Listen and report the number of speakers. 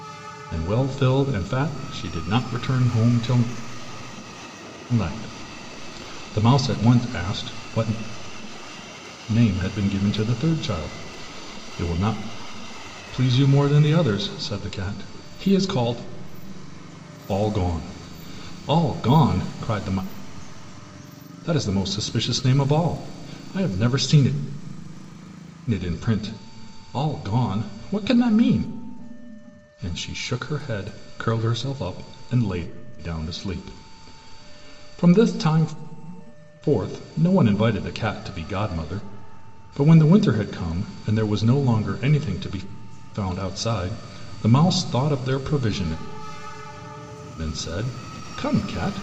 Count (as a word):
one